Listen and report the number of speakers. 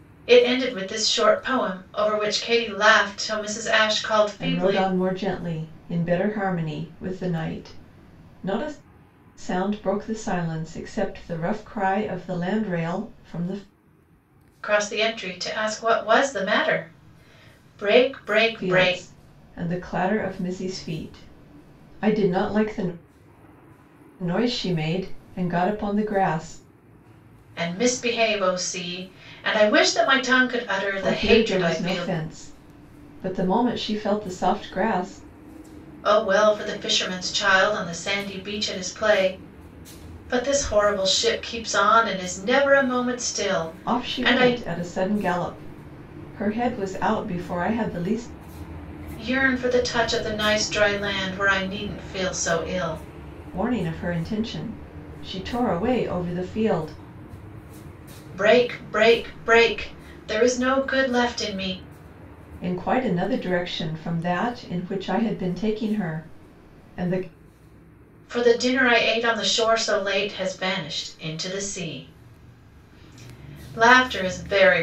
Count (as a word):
two